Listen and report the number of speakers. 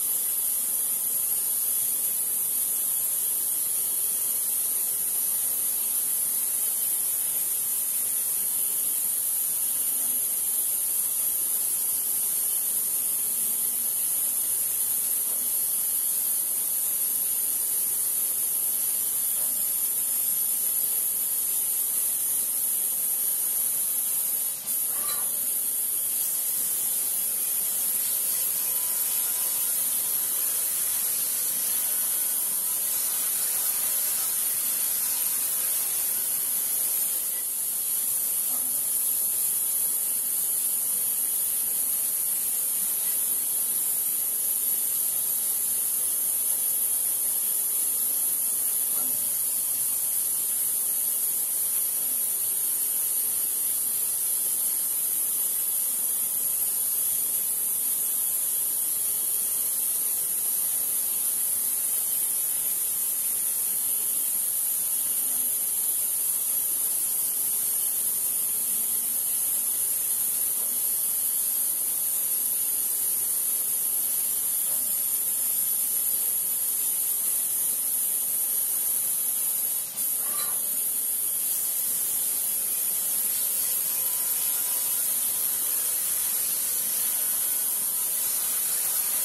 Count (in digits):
0